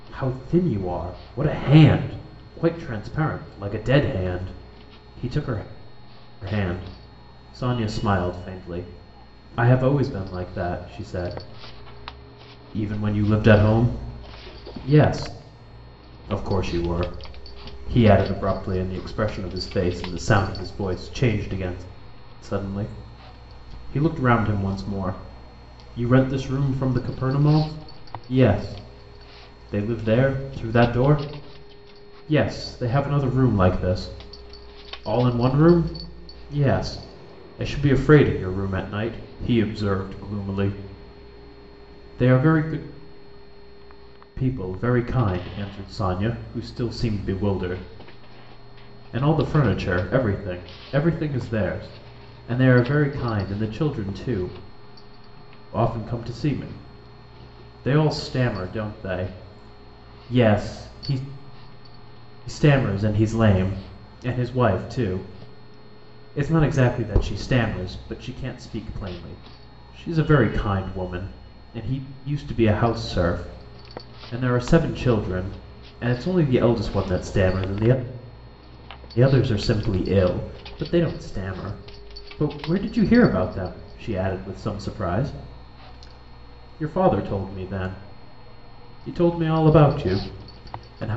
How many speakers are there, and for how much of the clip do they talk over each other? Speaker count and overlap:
1, no overlap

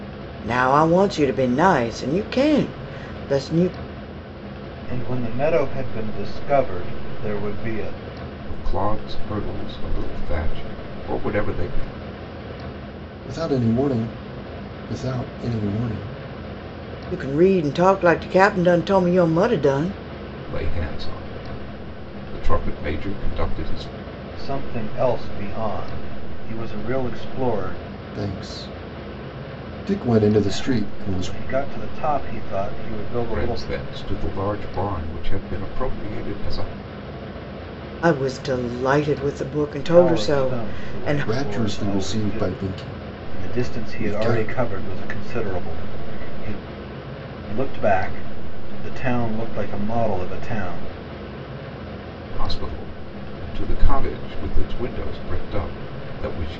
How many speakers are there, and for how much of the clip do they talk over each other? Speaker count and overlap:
4, about 10%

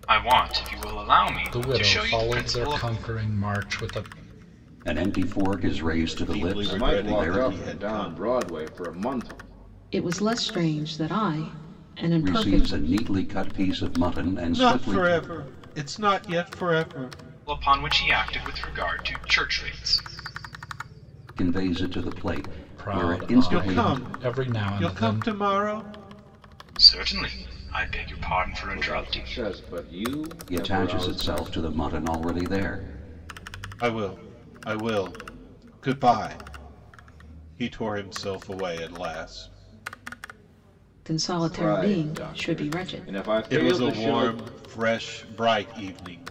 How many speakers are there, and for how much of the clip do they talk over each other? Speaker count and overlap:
6, about 25%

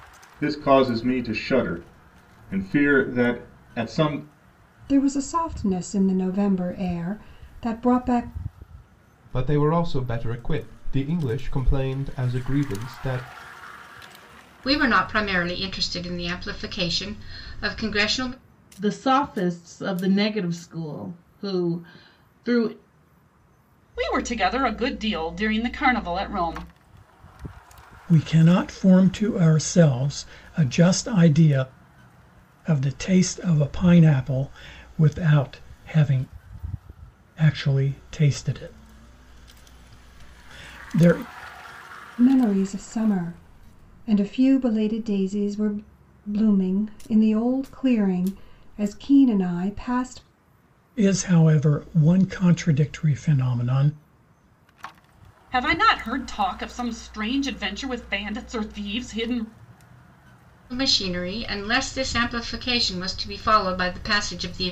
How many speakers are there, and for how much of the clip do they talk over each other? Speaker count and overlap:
7, no overlap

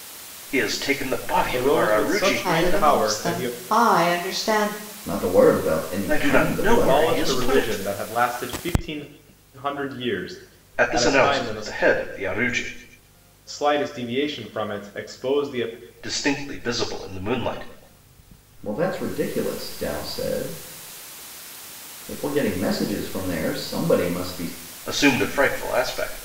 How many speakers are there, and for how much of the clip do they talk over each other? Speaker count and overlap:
4, about 18%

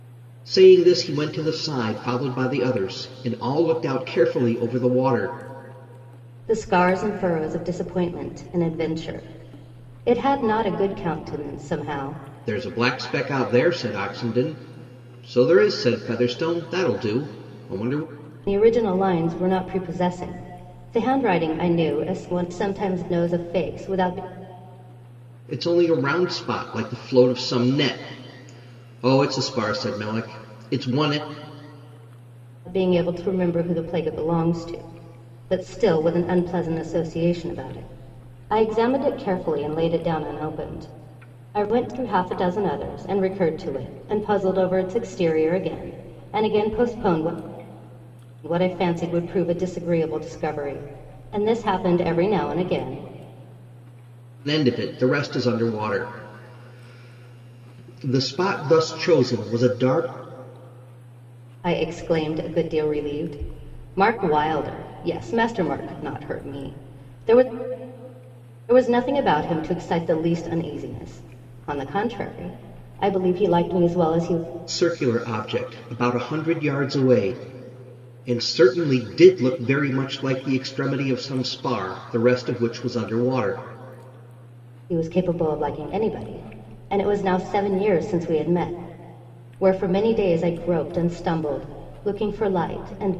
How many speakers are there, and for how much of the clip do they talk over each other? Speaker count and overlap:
2, no overlap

